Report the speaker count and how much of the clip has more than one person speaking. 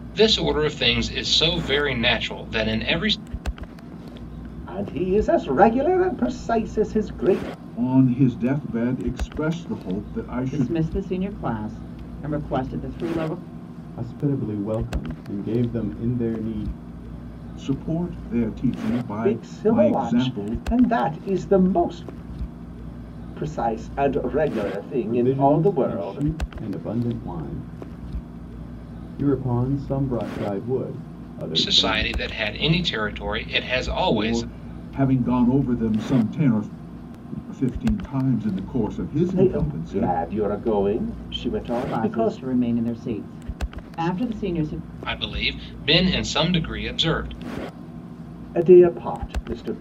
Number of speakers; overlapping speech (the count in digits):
5, about 11%